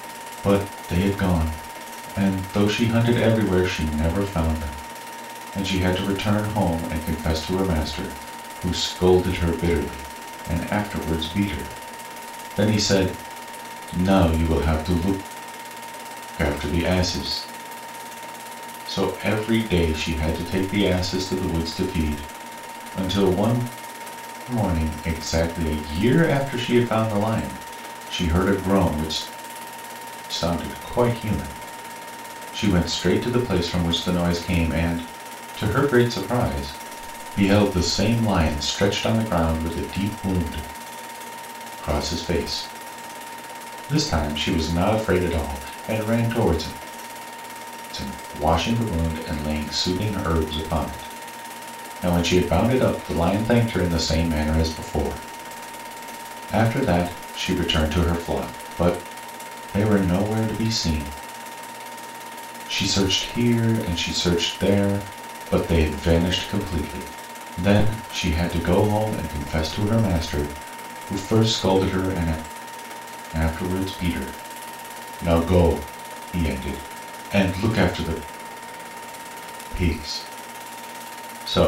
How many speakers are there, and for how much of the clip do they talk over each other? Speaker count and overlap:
1, no overlap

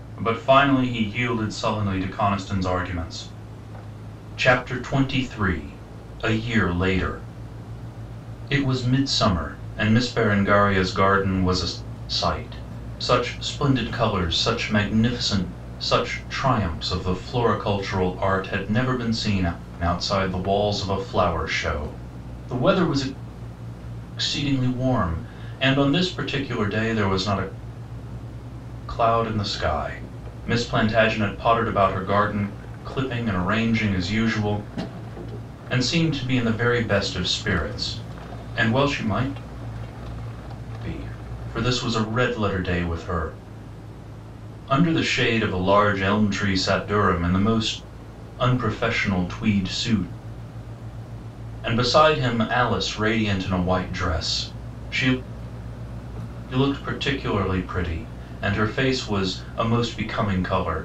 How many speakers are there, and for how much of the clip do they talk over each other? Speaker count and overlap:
1, no overlap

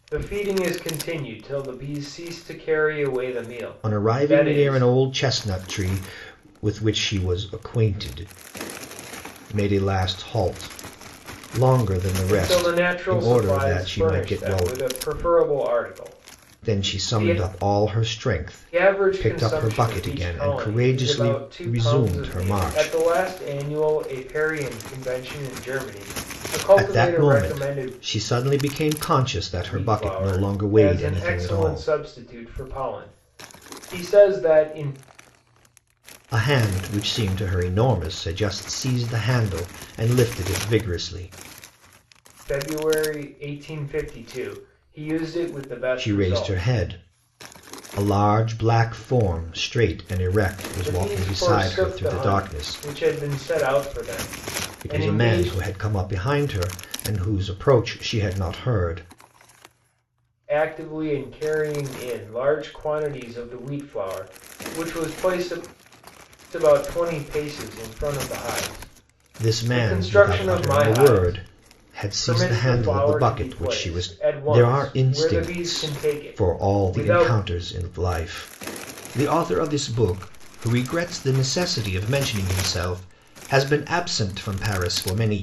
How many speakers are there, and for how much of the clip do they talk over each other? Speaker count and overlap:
2, about 26%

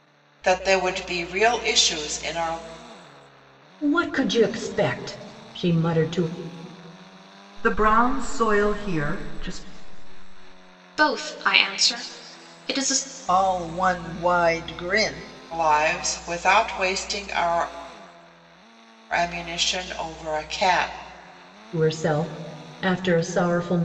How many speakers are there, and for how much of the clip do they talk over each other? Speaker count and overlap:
5, no overlap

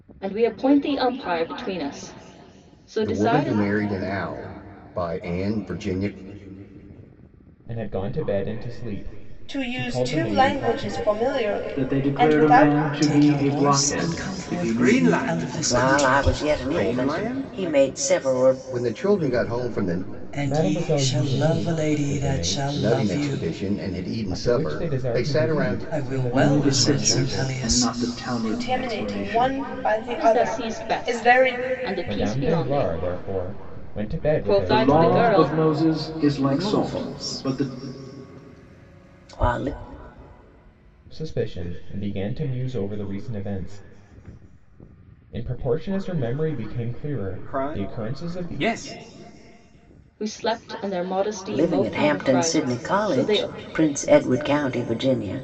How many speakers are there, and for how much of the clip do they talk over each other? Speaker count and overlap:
8, about 46%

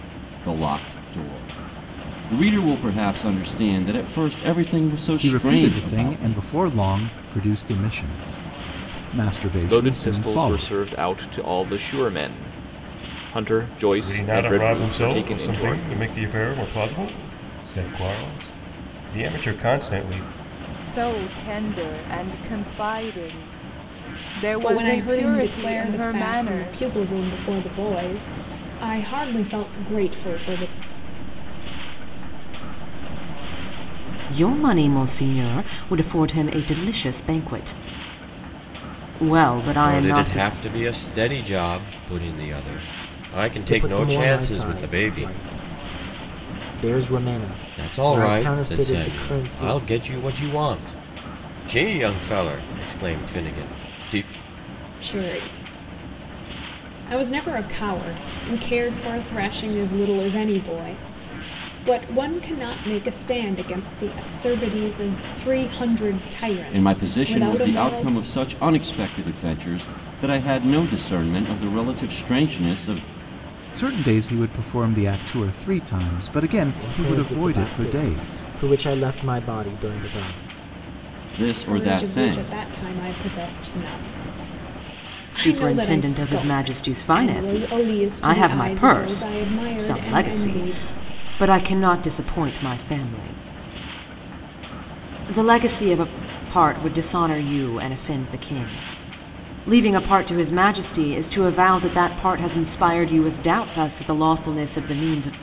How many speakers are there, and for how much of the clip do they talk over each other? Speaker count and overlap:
10, about 23%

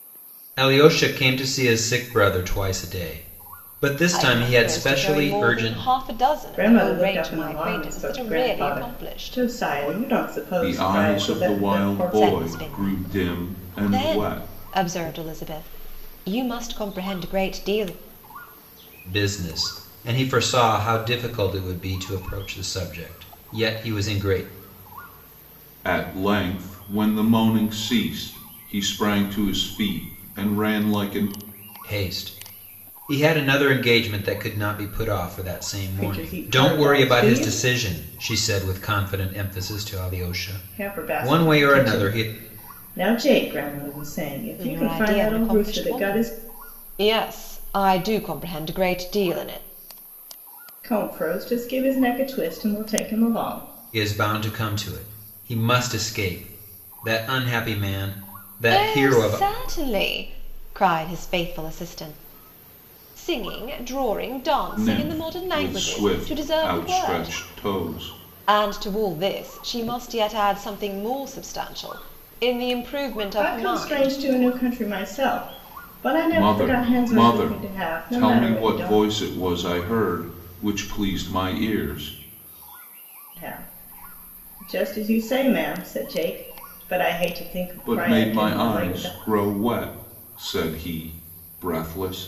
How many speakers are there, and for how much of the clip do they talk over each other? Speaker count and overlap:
4, about 24%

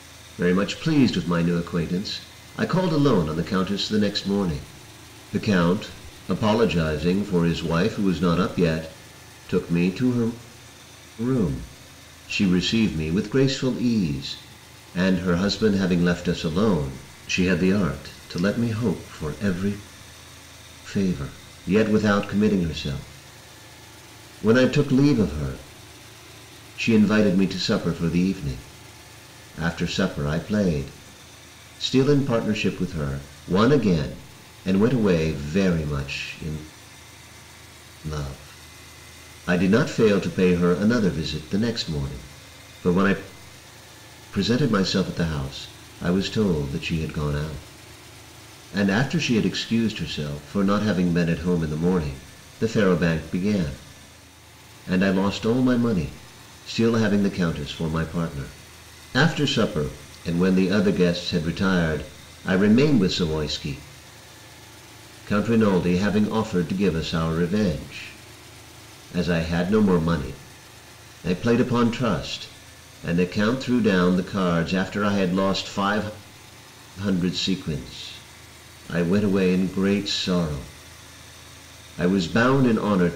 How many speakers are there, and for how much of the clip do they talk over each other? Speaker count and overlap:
1, no overlap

